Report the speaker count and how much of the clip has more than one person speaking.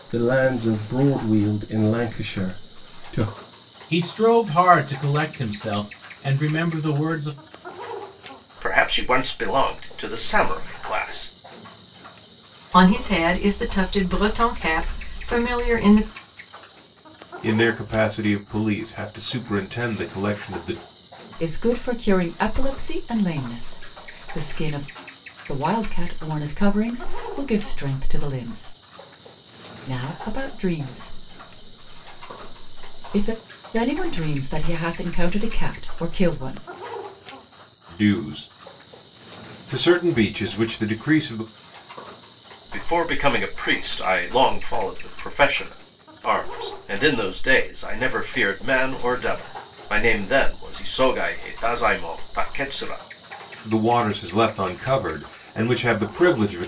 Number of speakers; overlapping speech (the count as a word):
six, no overlap